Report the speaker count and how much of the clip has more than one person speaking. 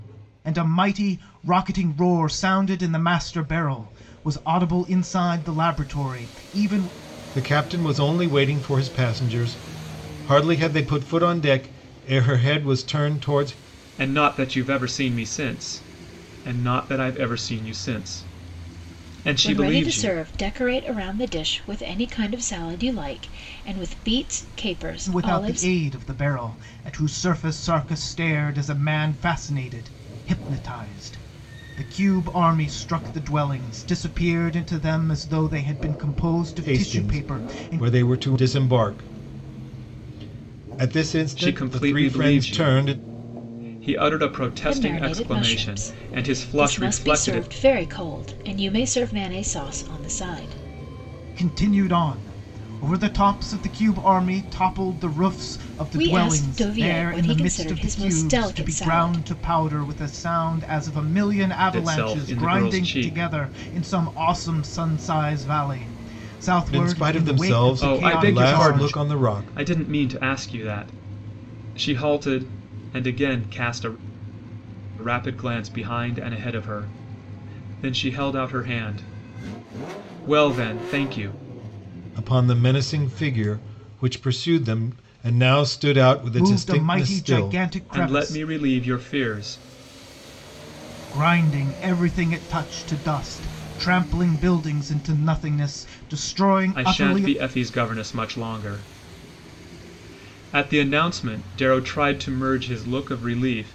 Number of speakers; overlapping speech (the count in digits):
4, about 17%